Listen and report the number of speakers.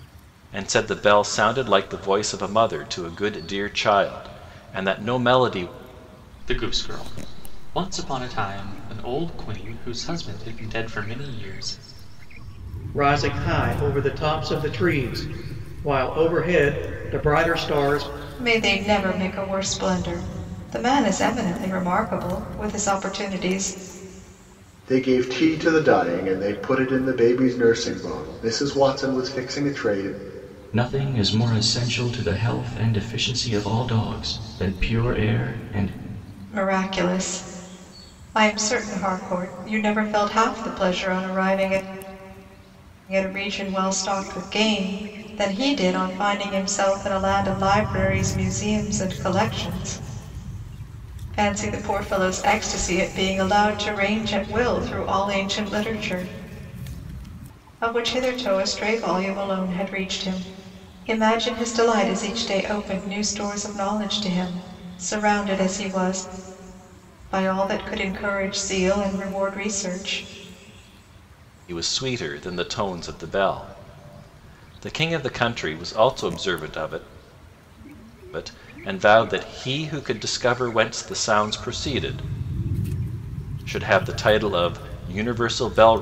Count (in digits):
6